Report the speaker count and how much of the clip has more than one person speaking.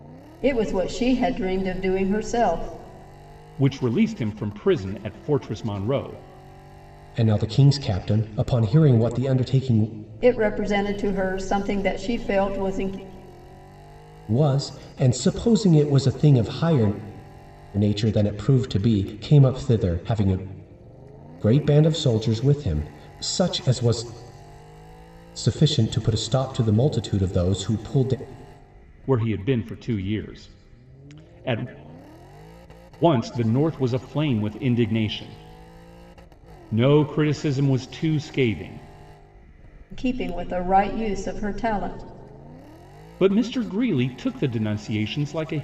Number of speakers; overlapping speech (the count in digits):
3, no overlap